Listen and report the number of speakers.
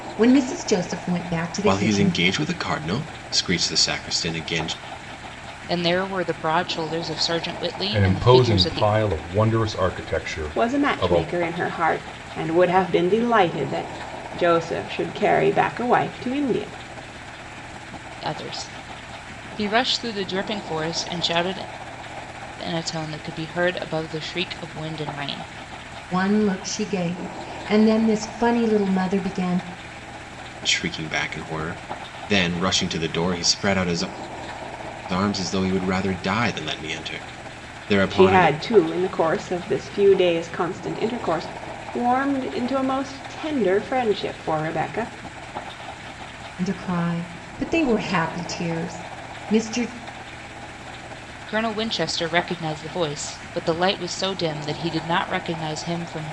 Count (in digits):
5